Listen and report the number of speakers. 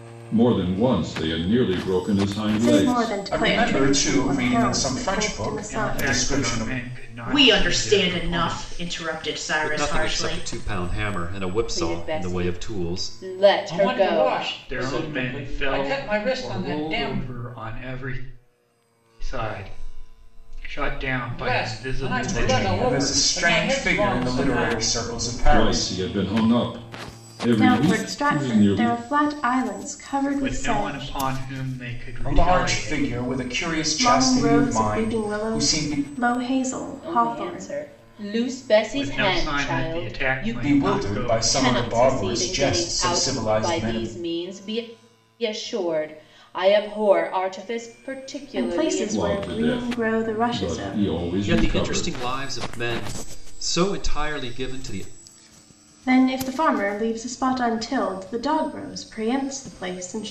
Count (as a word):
eight